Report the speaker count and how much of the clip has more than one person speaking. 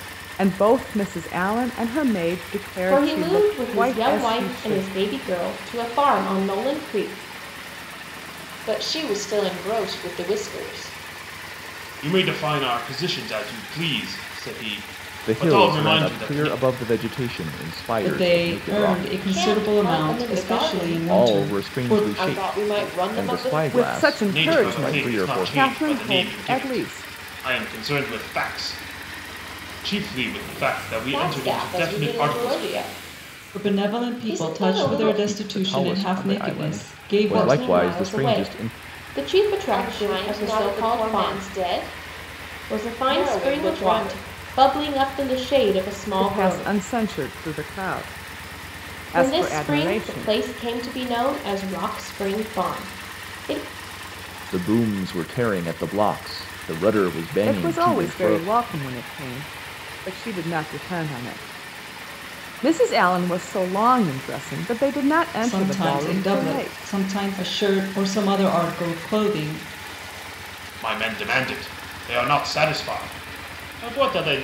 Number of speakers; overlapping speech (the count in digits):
6, about 37%